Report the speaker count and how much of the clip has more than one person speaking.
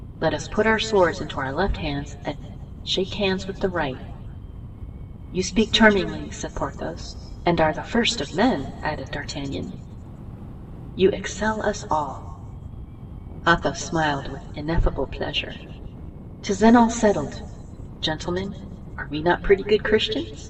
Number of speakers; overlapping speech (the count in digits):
1, no overlap